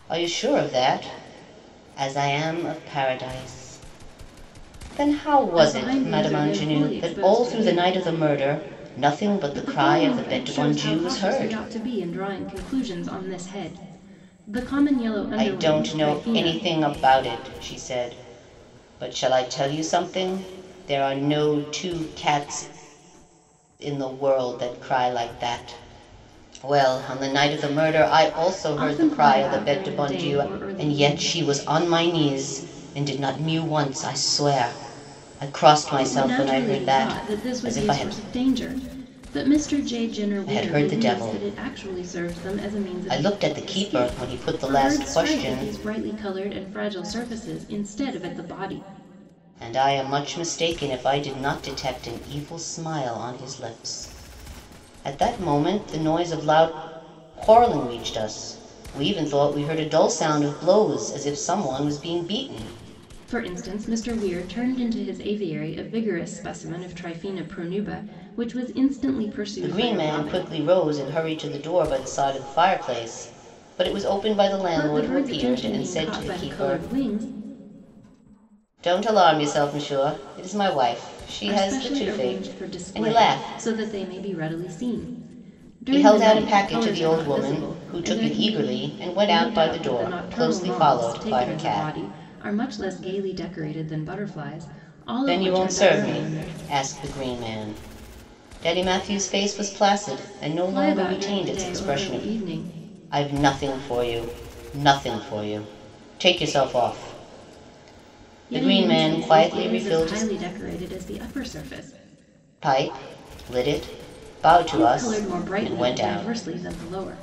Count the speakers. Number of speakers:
2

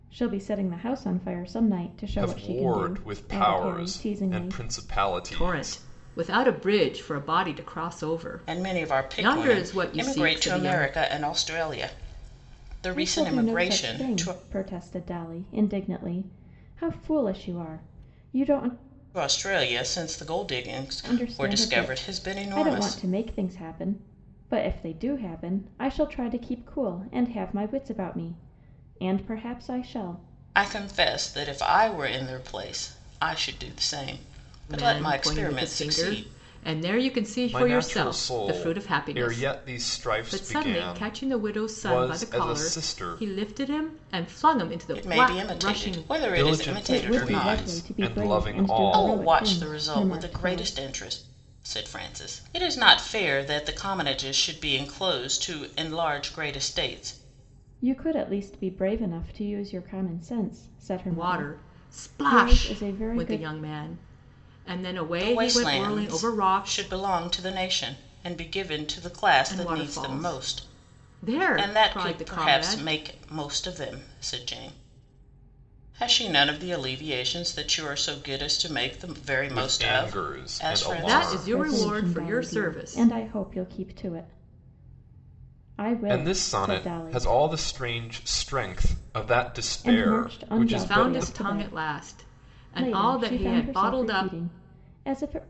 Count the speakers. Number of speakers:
4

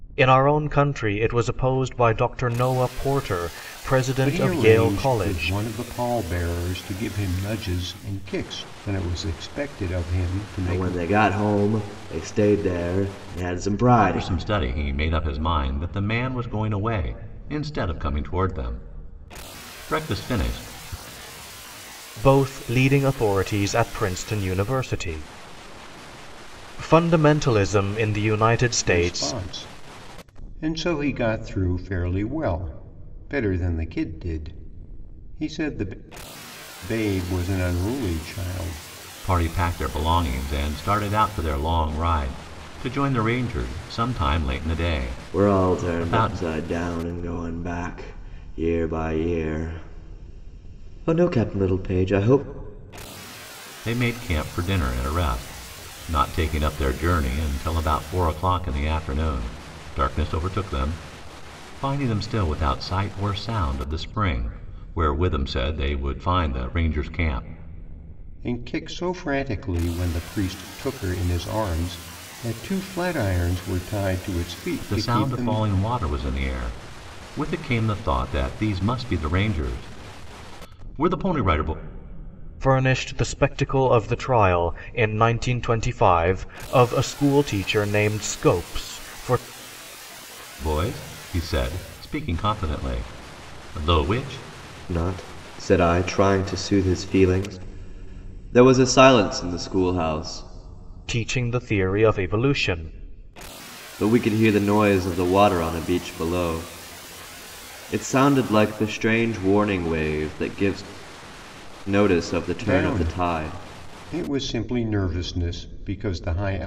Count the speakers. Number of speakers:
4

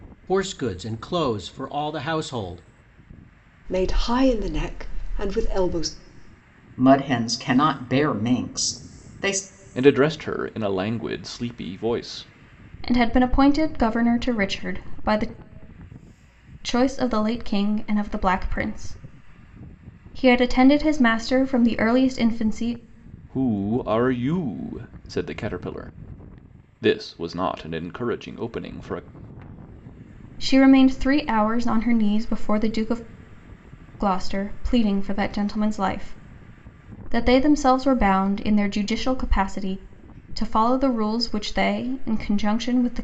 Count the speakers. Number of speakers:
5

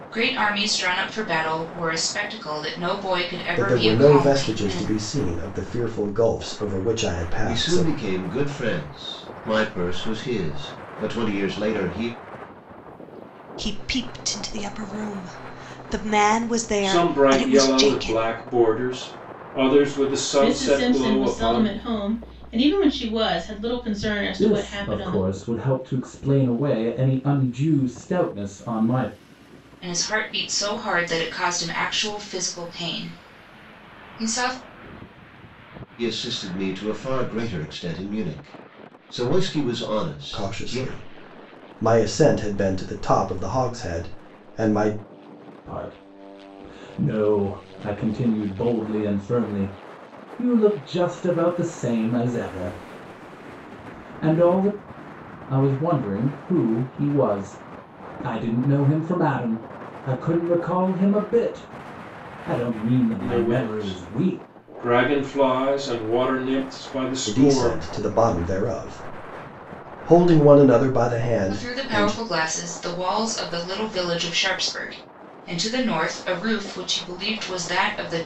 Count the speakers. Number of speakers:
7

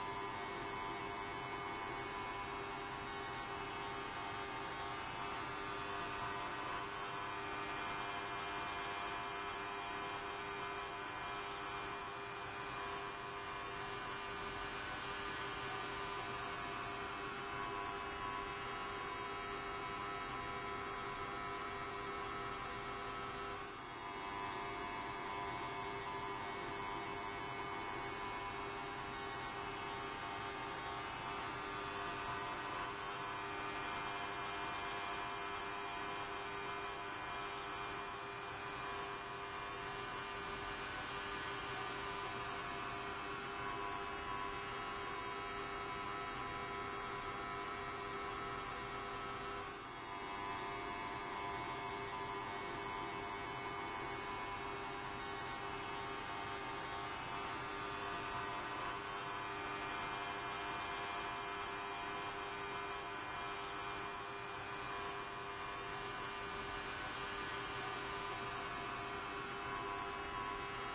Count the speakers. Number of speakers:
0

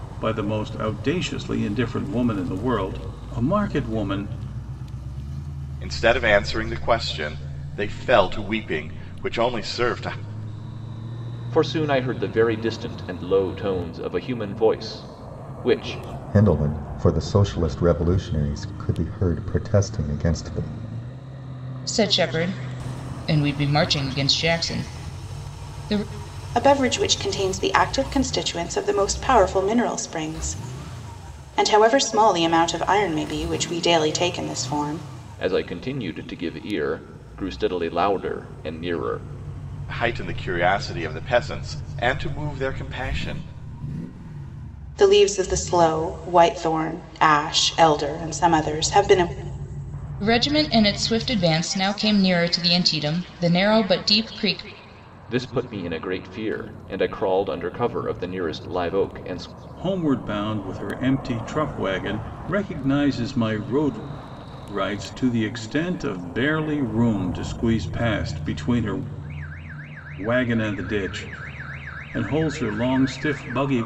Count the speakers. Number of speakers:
6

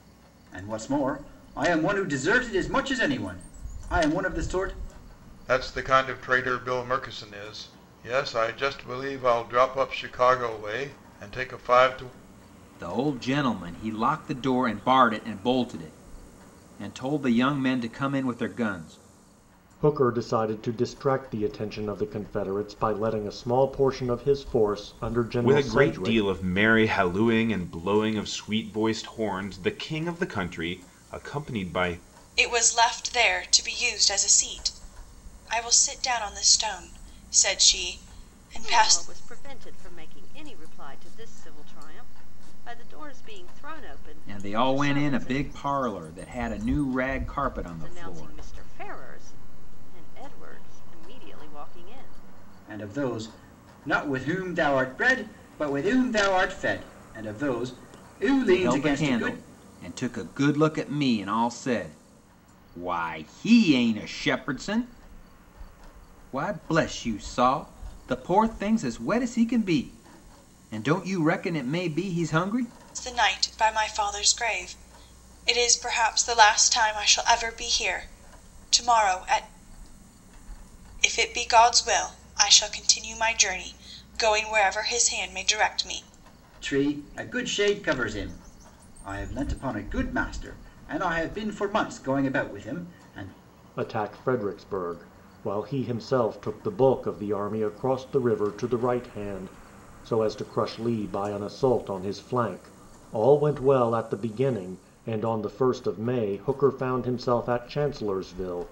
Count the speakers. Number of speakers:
7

